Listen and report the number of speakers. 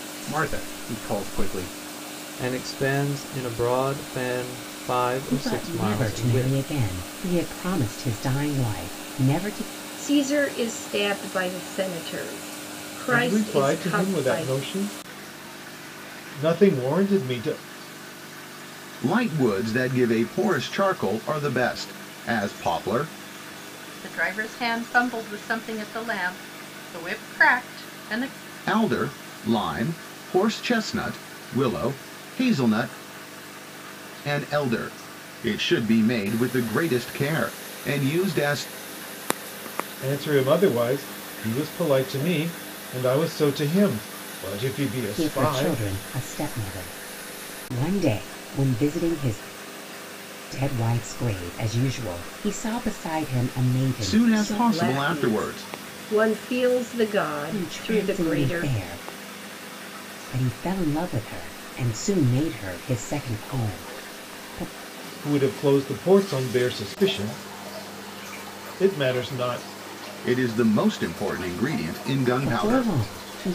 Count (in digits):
7